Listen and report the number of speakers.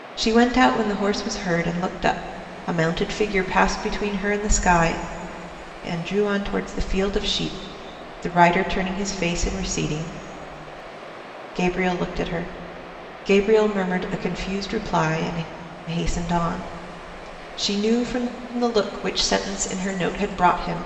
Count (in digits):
1